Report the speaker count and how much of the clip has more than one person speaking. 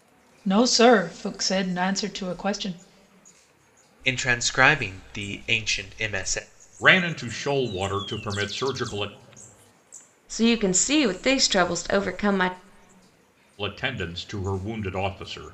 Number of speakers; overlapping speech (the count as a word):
four, no overlap